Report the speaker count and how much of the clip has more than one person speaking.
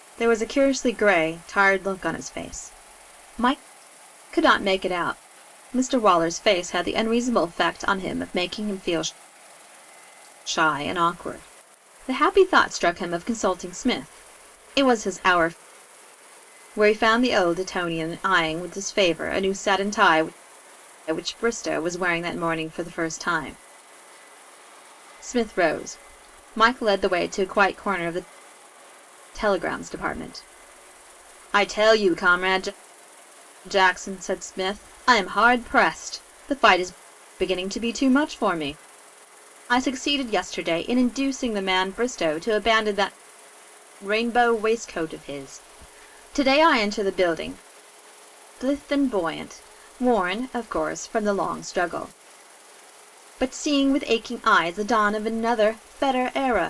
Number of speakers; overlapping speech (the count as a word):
one, no overlap